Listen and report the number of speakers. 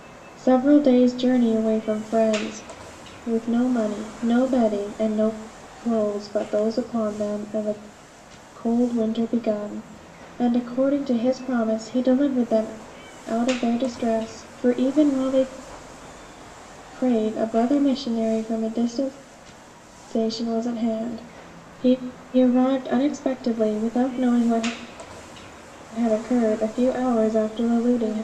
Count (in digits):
1